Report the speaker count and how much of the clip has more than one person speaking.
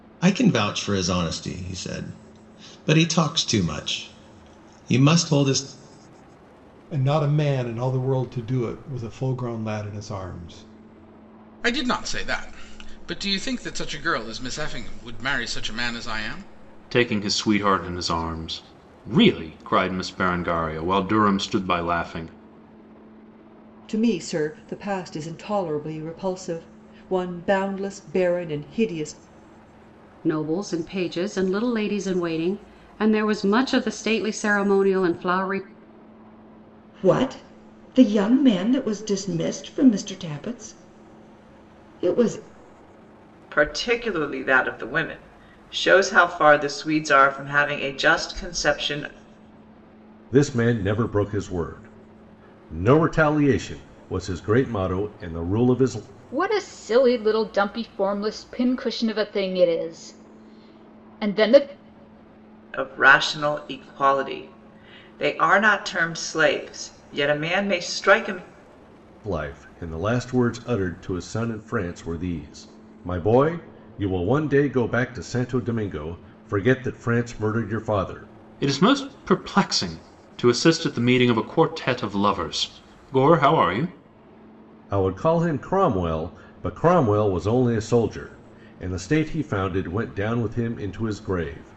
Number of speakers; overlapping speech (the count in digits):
10, no overlap